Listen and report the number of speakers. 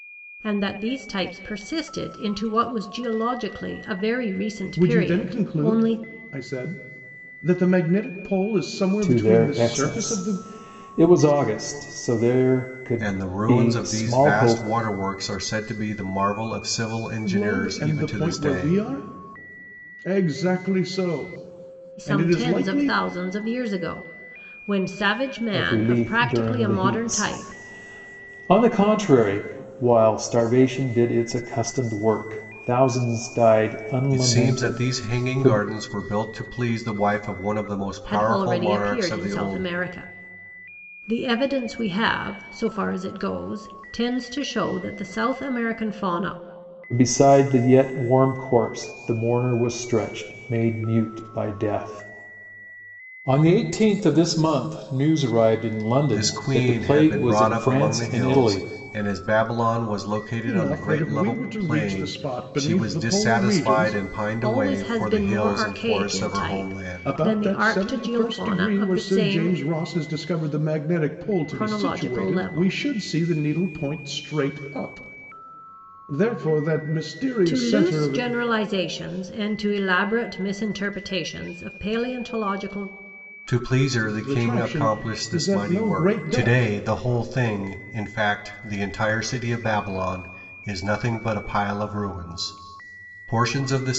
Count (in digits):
4